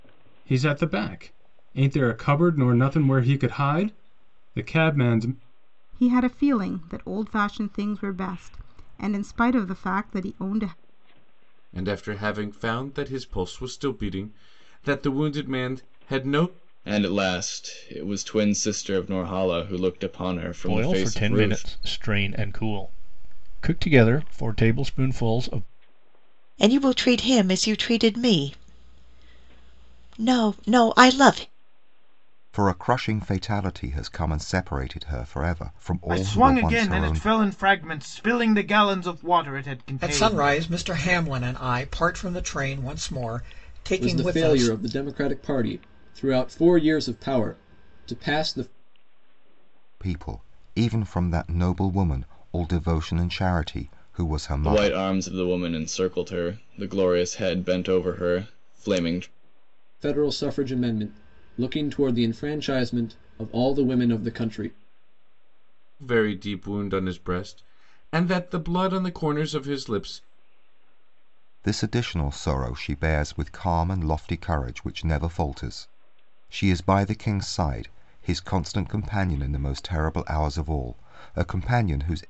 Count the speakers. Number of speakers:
ten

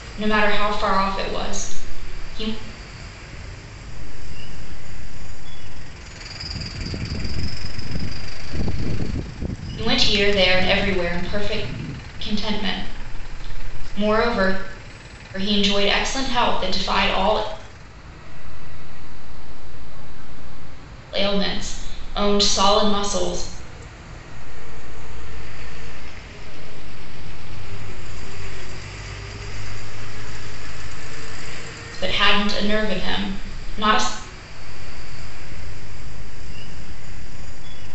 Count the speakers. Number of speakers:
two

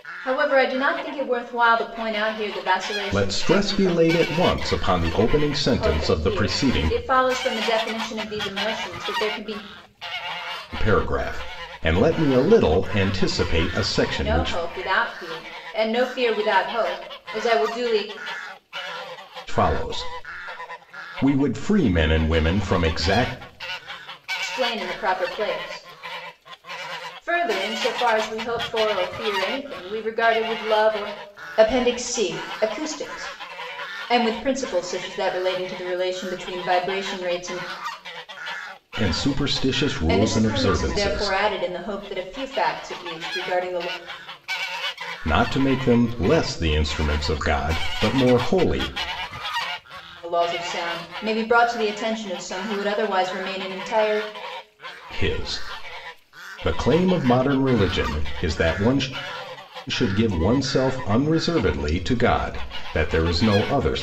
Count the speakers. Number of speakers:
two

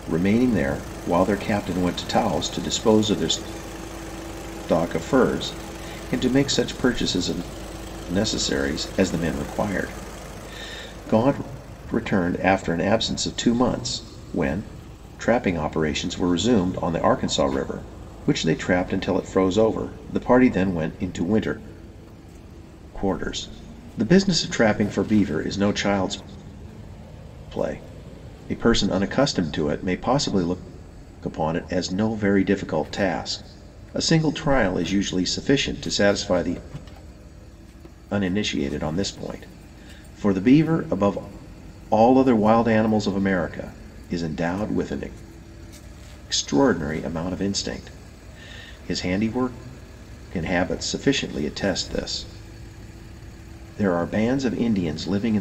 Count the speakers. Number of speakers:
one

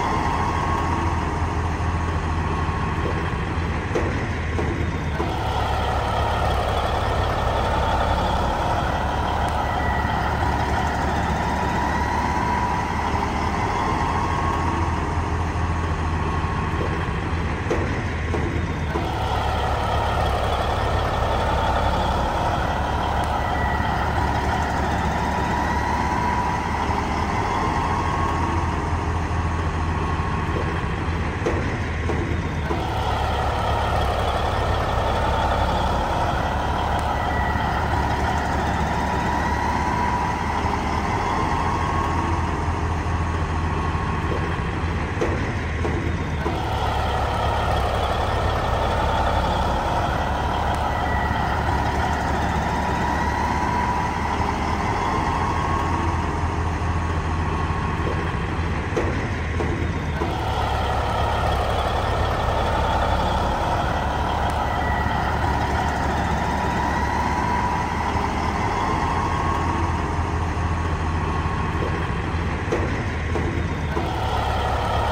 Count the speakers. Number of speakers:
zero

